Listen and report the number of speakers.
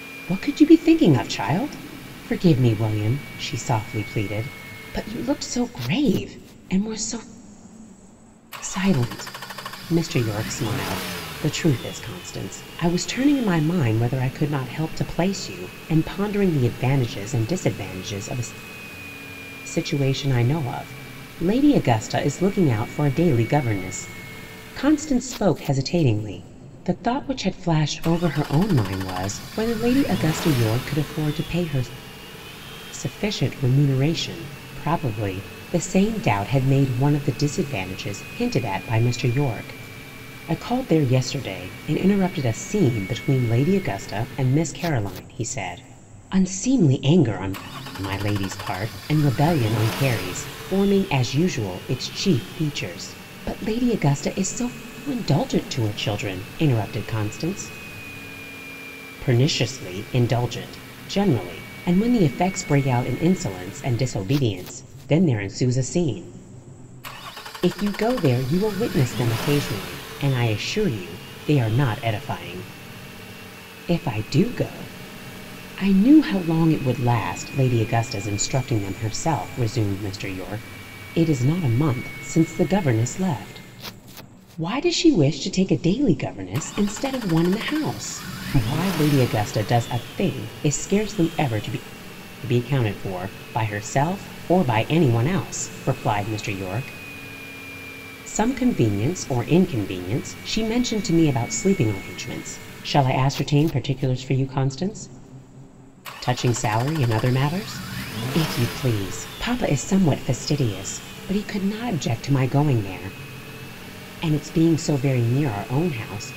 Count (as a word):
one